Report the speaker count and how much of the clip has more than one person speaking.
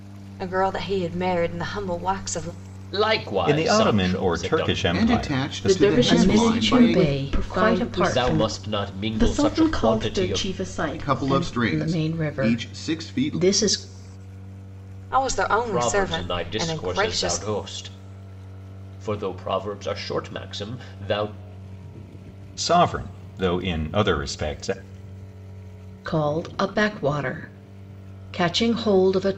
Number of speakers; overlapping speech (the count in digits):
6, about 36%